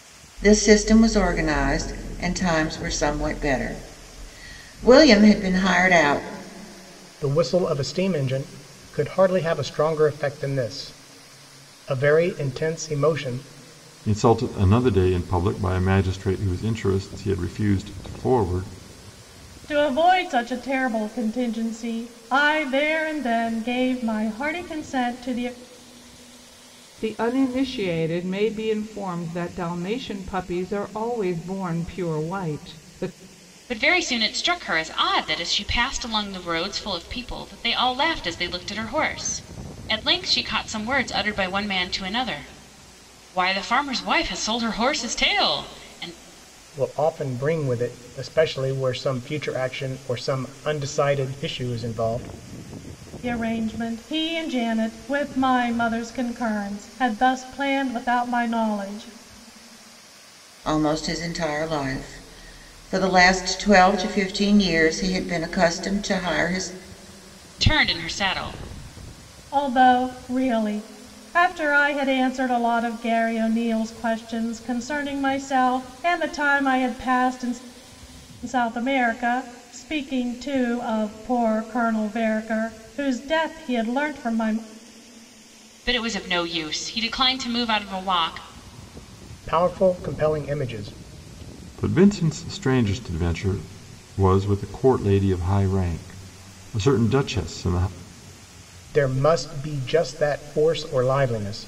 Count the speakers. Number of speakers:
6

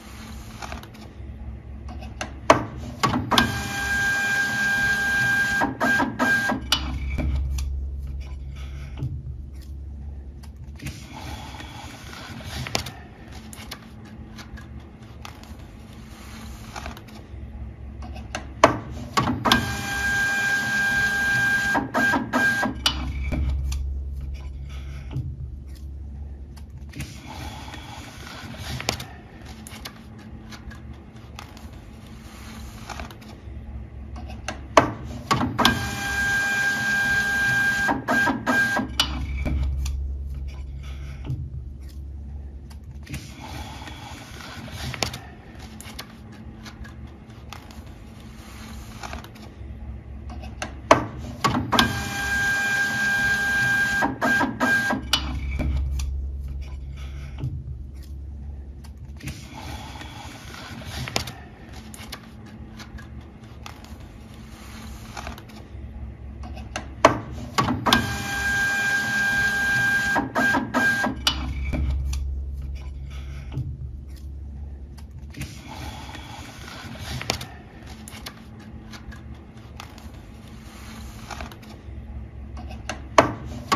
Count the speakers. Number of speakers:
0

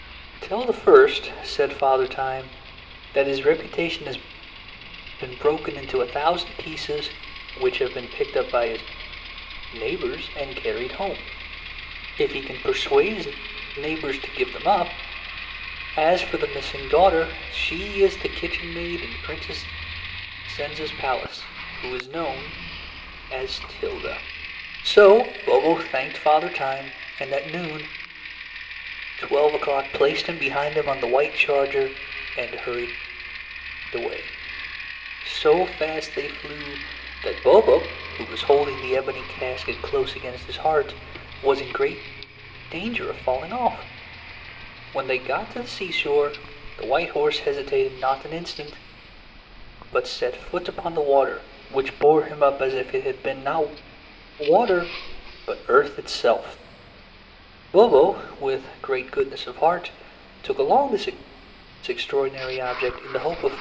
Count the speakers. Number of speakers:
1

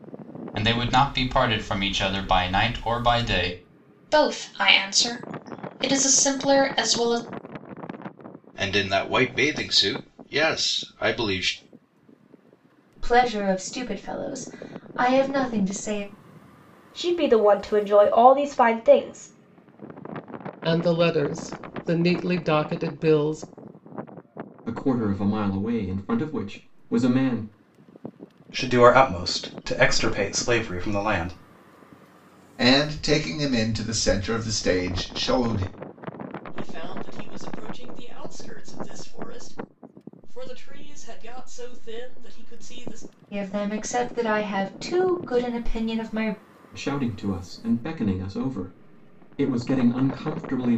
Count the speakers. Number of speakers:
10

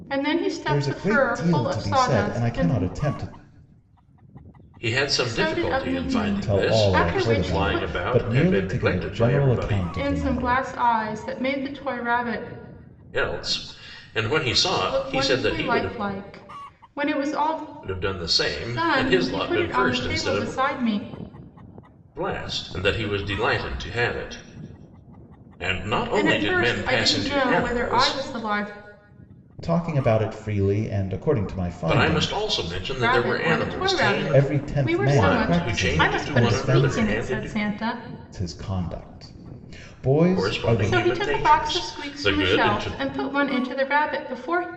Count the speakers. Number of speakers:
3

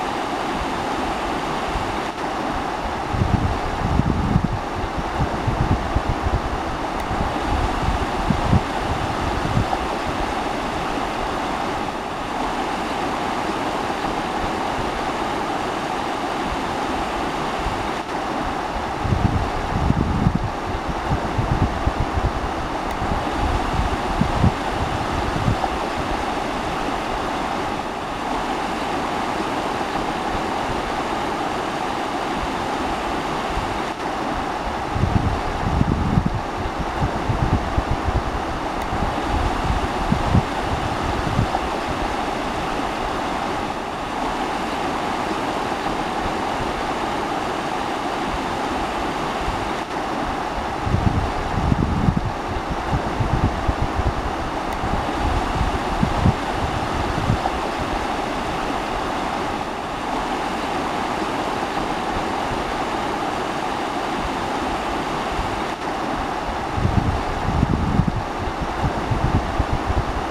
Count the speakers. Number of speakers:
0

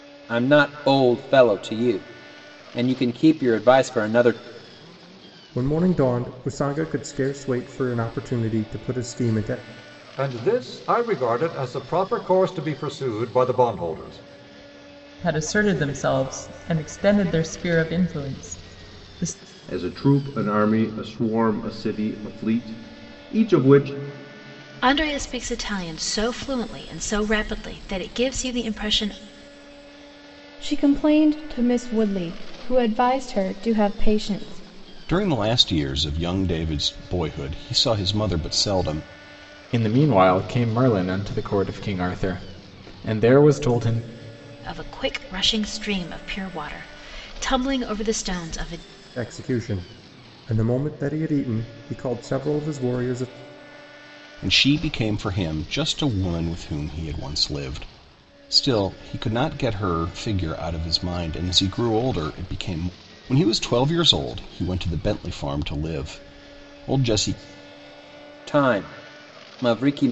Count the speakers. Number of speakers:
9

